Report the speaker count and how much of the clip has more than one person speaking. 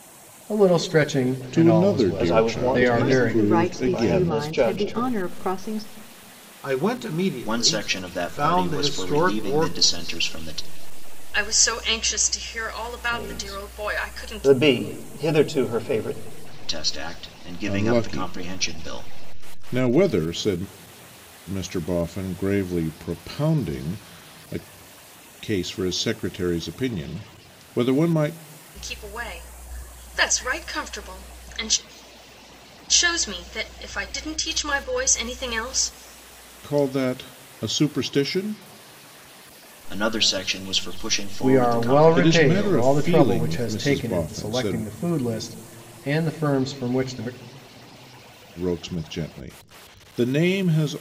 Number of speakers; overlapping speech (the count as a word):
seven, about 24%